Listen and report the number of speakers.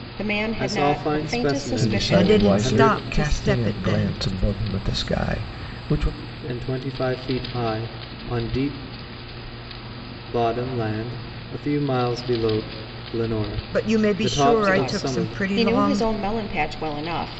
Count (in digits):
4